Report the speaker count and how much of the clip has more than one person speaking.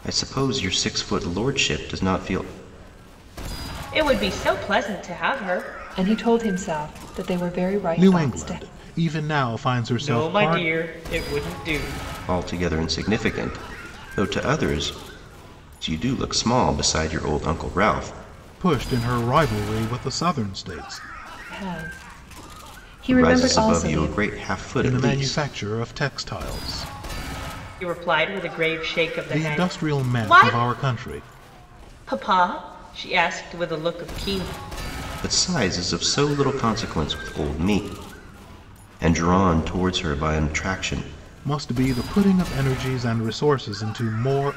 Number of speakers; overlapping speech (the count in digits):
4, about 11%